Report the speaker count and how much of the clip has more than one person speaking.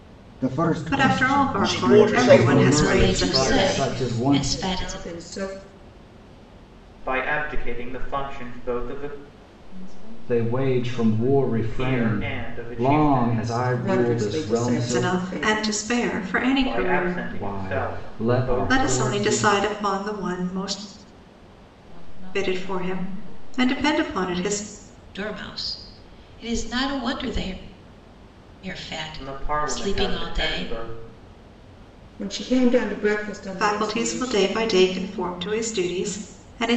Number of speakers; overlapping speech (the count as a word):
eight, about 42%